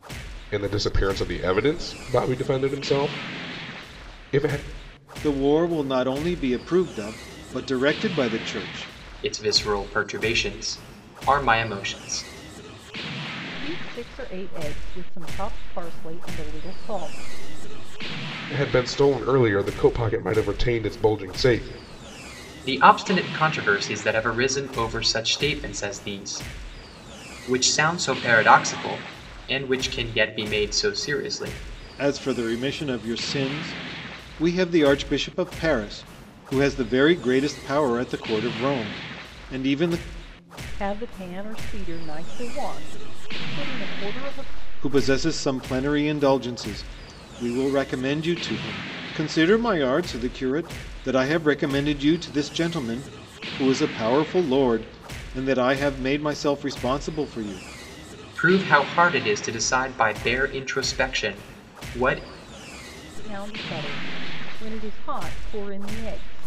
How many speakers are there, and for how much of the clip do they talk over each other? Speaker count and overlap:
four, no overlap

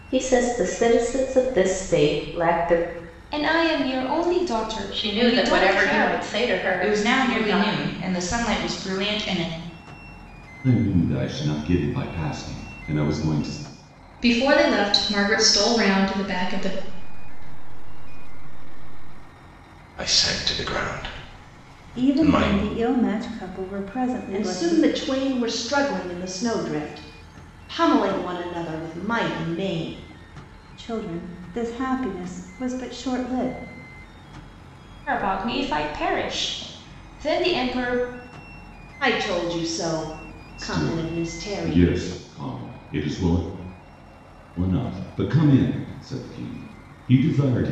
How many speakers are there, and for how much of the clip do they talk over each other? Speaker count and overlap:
ten, about 11%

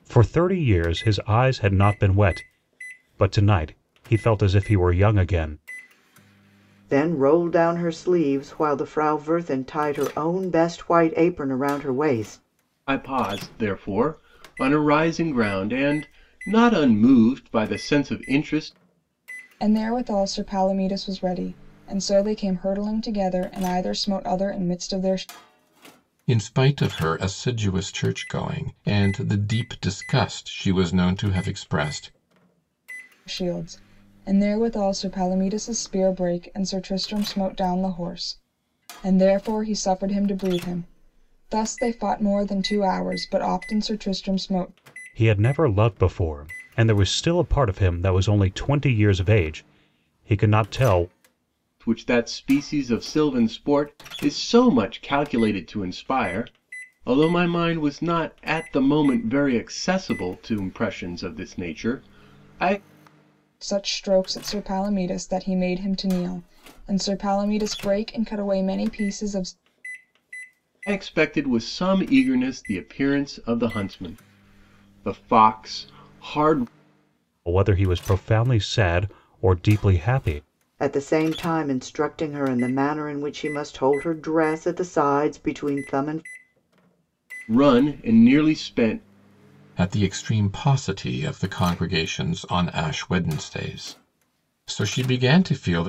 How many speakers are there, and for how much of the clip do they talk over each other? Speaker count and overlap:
five, no overlap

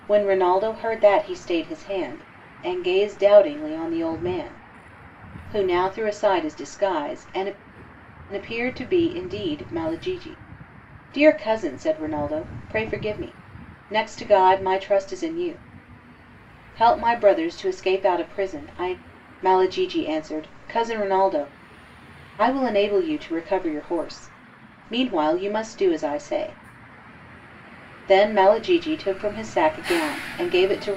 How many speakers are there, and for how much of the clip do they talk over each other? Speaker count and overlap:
one, no overlap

